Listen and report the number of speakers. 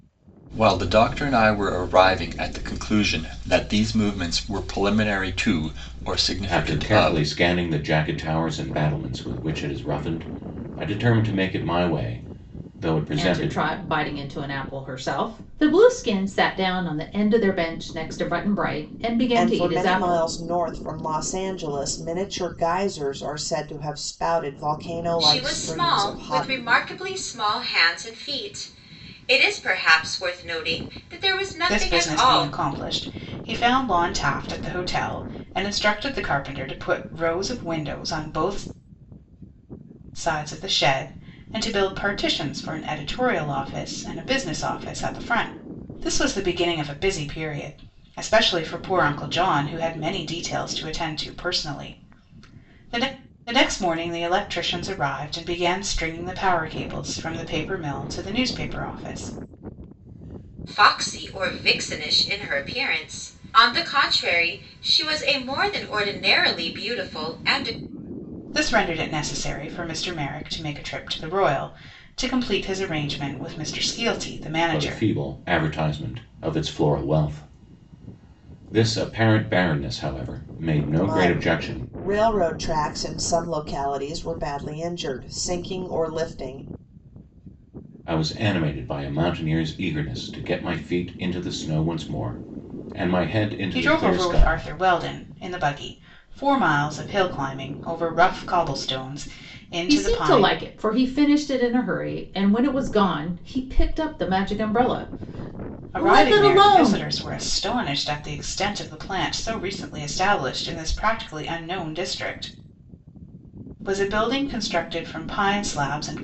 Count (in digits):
6